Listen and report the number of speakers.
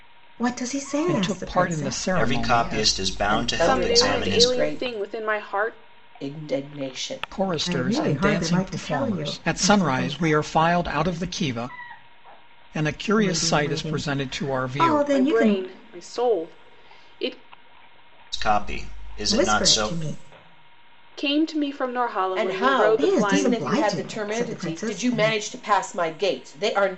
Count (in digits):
5